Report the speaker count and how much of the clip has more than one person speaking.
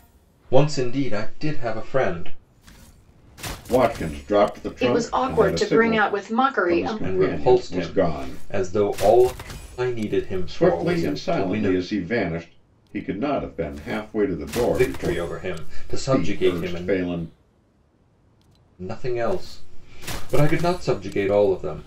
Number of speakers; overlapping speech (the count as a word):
three, about 28%